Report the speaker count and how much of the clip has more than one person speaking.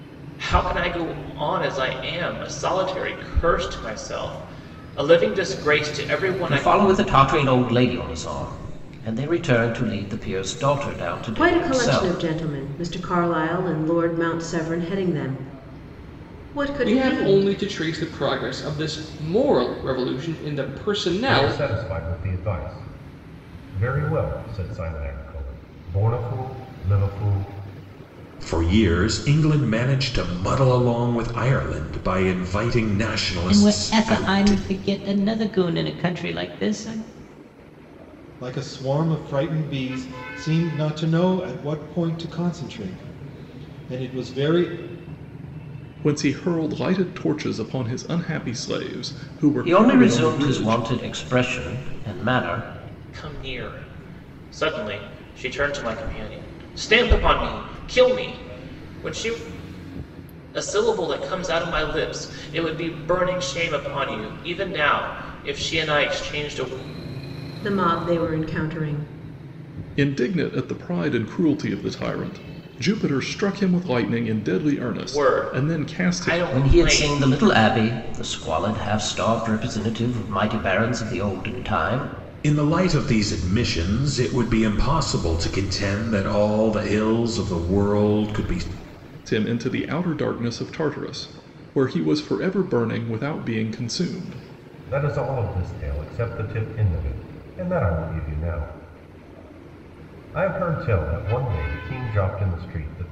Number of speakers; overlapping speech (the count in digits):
9, about 7%